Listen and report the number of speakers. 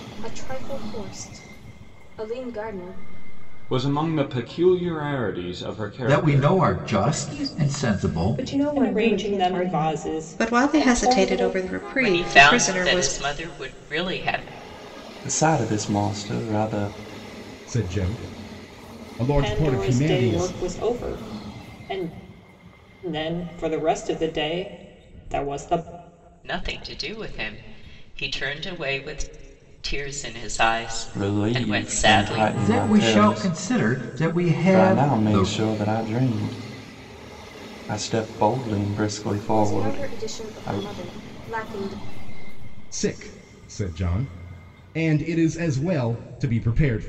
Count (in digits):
9